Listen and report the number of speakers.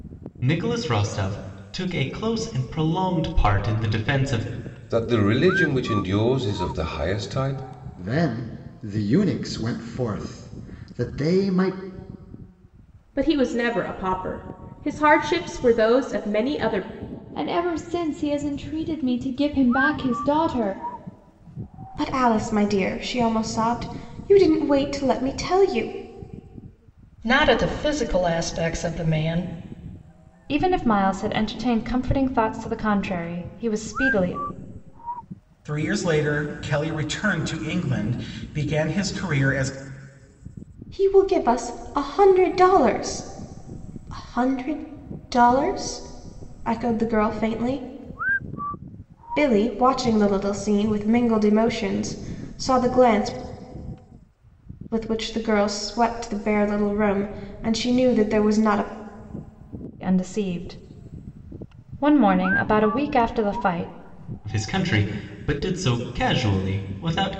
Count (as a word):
nine